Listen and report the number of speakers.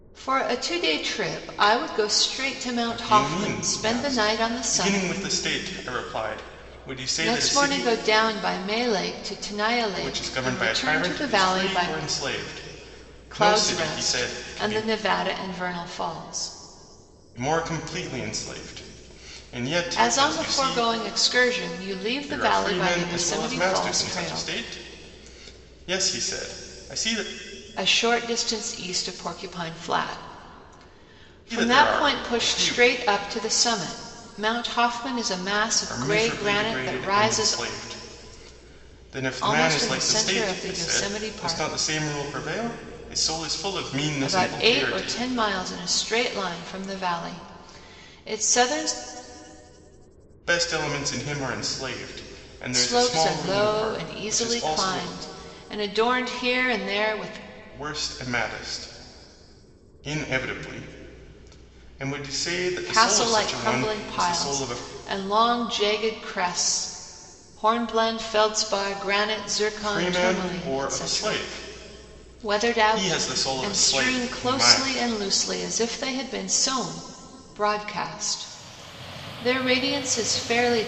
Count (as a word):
two